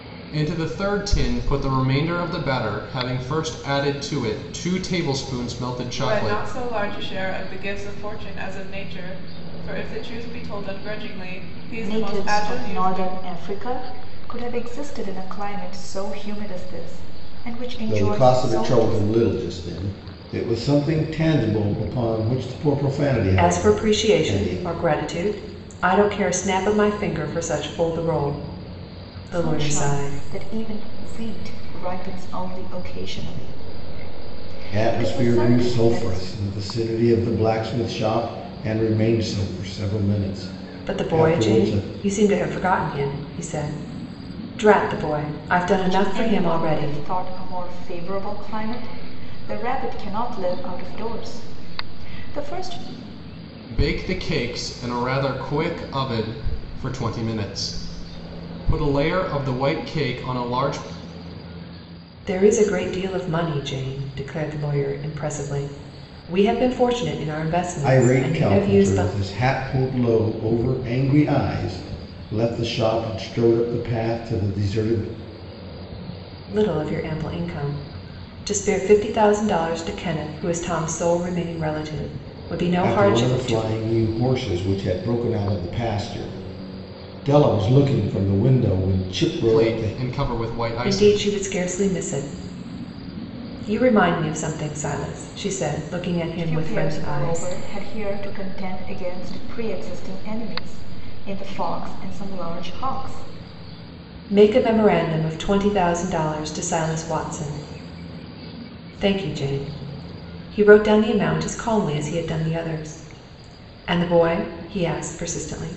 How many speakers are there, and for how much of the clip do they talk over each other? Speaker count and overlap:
five, about 12%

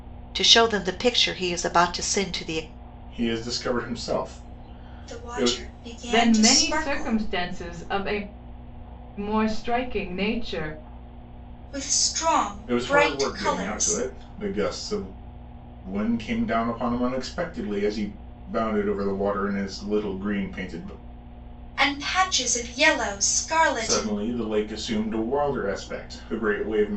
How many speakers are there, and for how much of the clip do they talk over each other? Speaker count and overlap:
four, about 12%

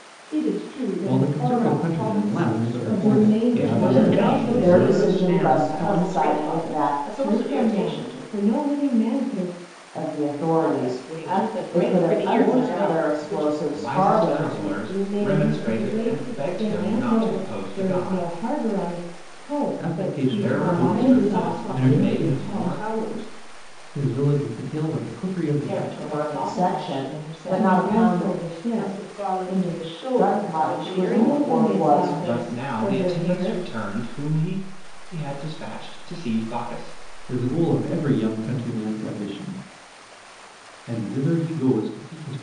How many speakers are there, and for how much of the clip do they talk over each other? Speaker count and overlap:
nine, about 60%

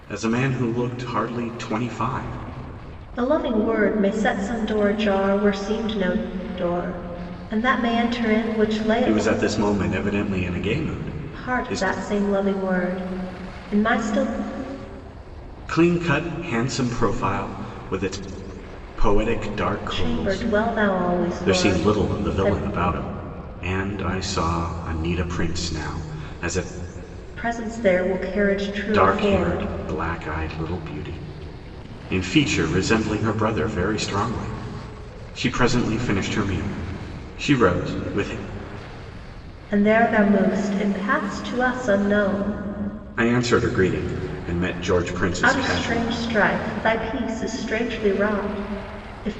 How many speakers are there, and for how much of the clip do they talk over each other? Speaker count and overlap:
two, about 9%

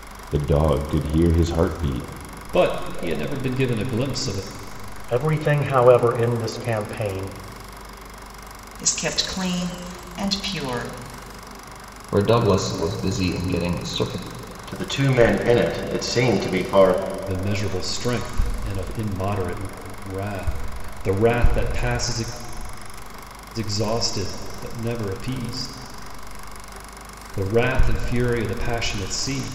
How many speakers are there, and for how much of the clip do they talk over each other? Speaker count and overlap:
six, no overlap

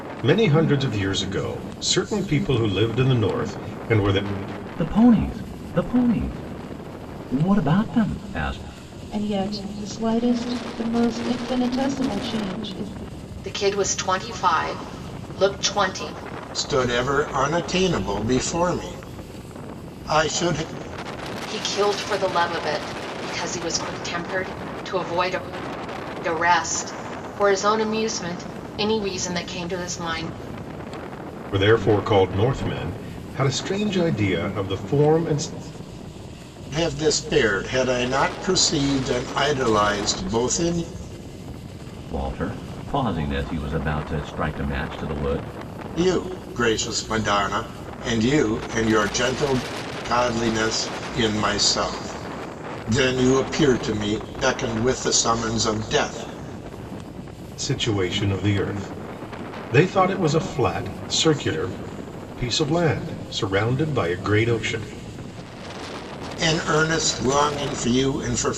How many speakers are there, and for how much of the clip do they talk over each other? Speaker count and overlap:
five, no overlap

